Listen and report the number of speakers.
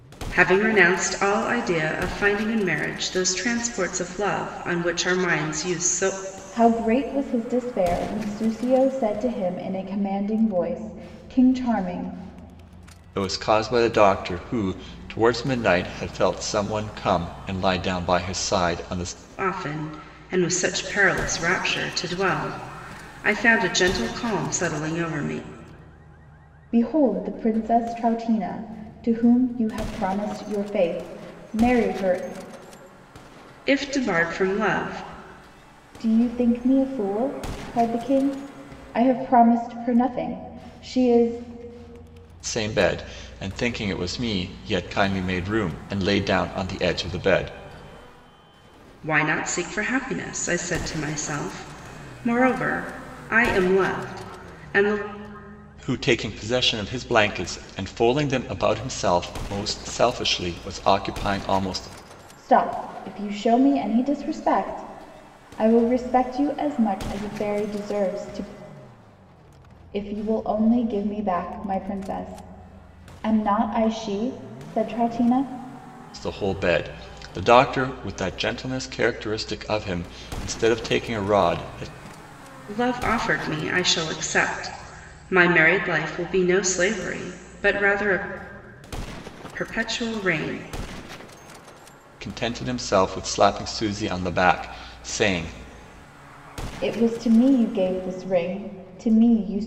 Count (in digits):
3